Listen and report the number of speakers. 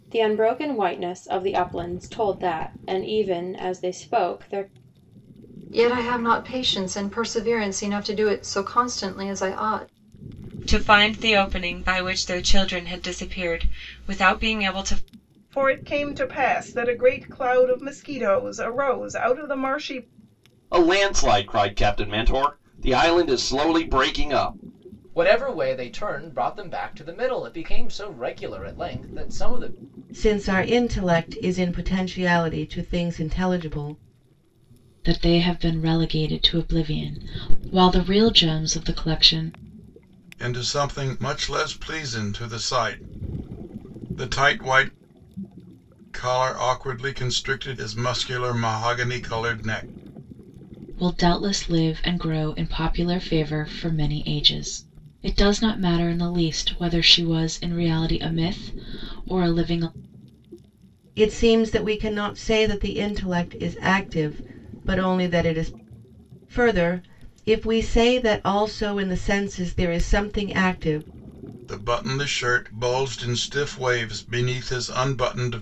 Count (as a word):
nine